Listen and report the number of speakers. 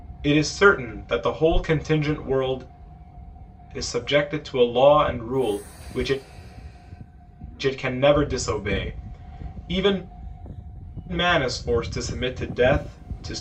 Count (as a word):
one